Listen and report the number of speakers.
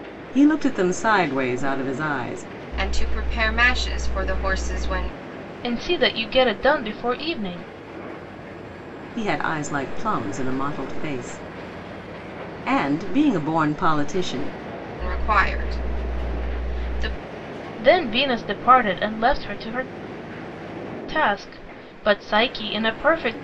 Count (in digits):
3